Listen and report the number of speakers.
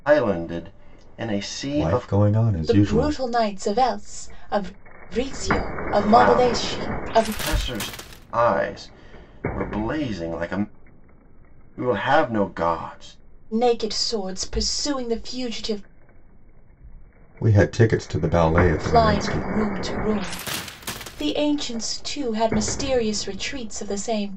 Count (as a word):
three